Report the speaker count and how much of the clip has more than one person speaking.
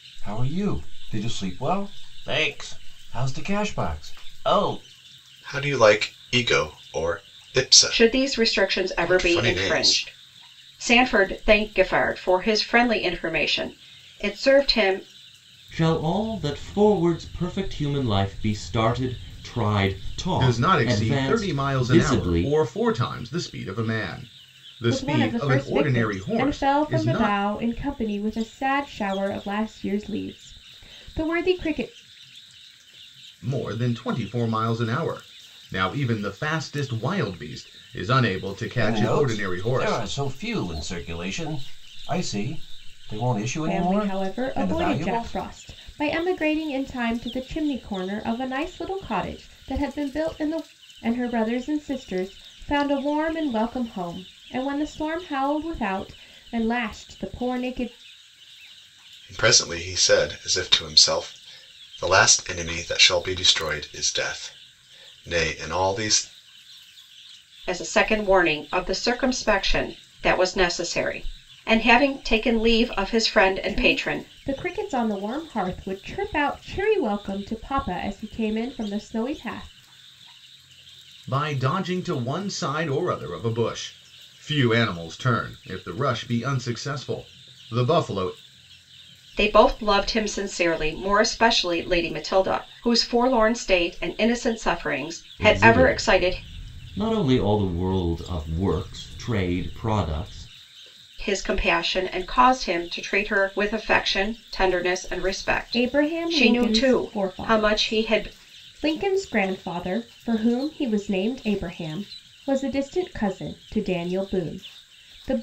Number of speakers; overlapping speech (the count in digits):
6, about 12%